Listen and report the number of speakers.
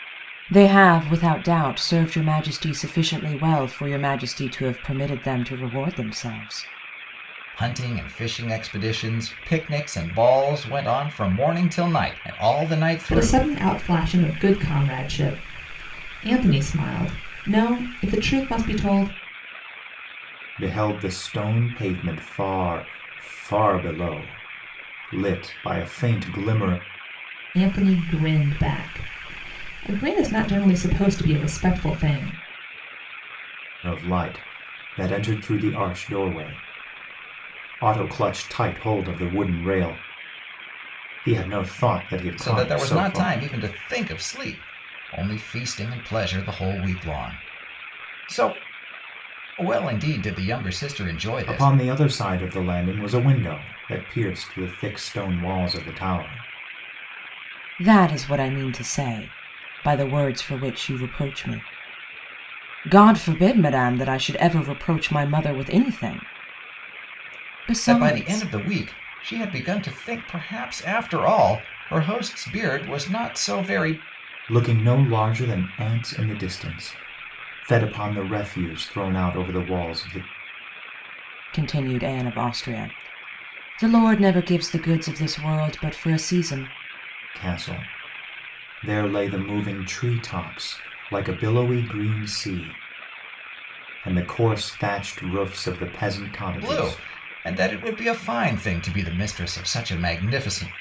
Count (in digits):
4